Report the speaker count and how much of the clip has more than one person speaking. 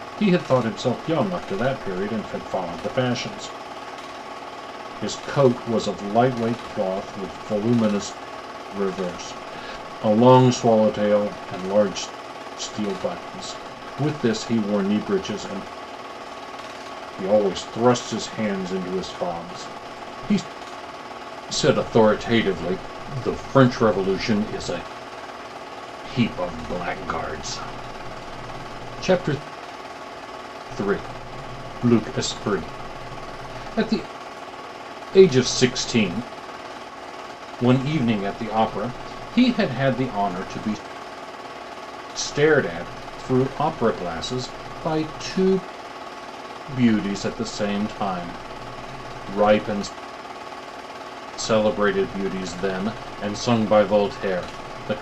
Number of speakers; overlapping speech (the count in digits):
1, no overlap